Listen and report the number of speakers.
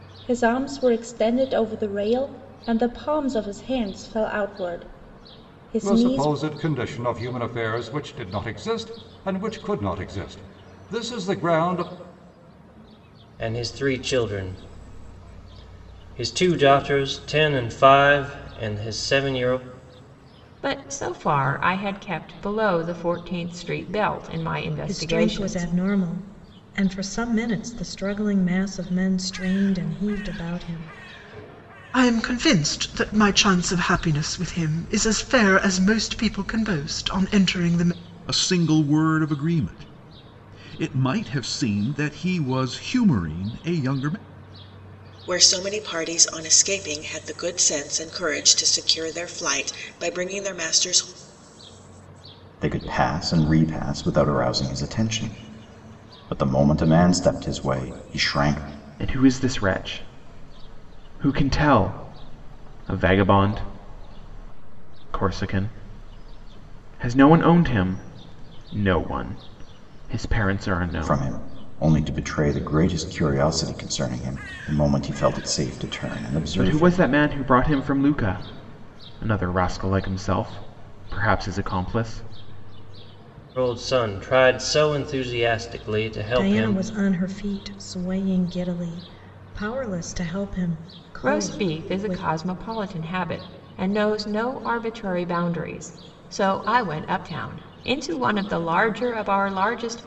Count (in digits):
10